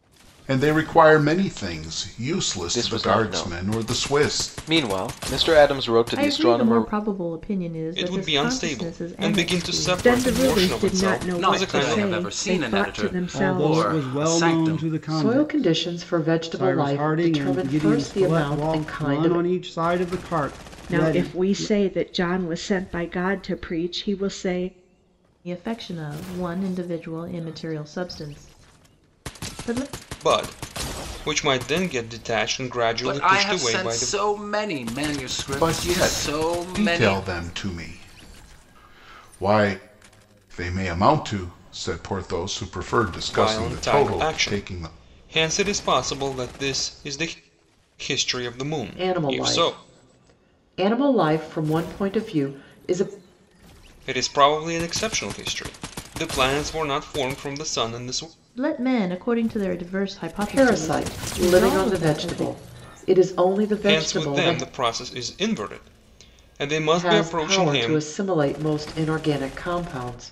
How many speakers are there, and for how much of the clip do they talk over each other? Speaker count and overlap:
8, about 34%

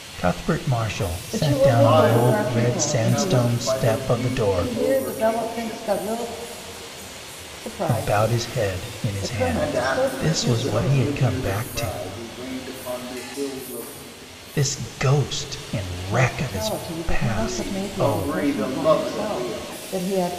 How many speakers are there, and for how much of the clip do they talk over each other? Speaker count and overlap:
3, about 57%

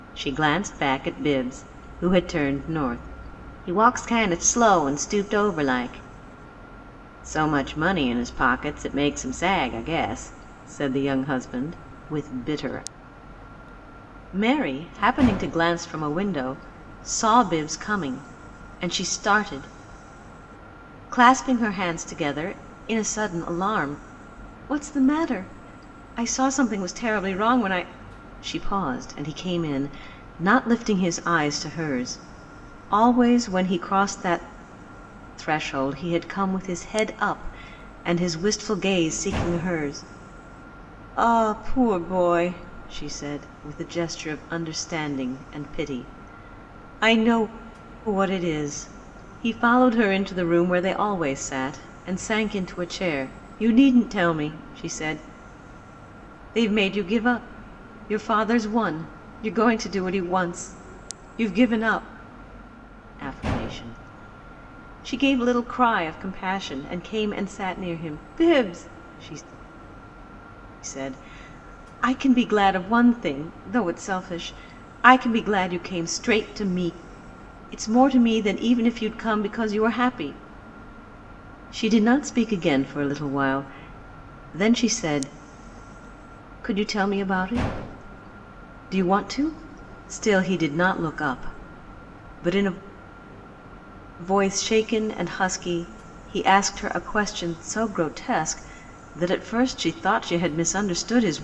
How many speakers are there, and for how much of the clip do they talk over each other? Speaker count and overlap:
1, no overlap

